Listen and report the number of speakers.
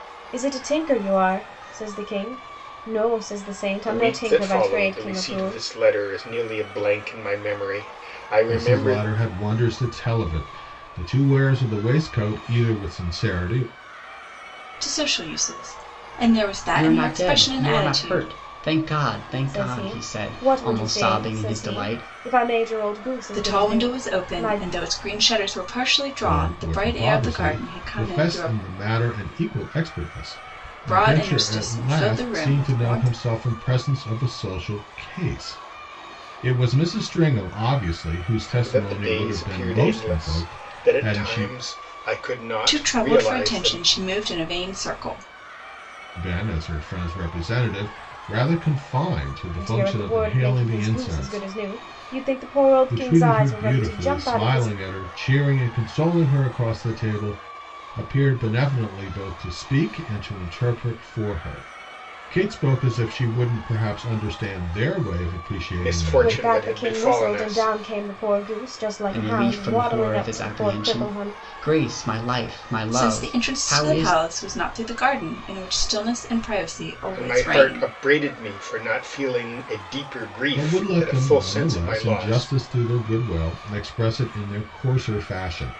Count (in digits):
5